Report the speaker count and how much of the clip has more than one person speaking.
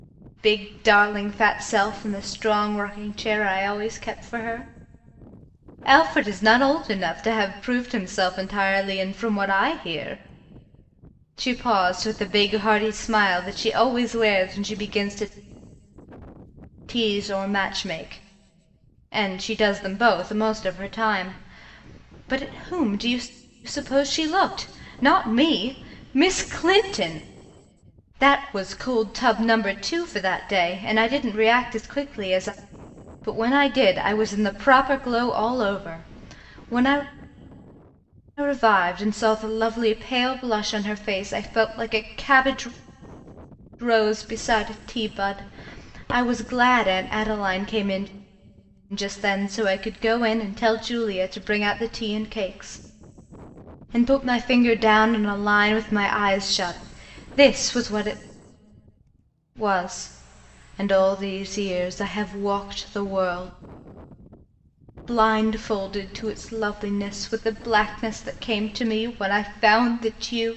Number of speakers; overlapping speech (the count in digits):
1, no overlap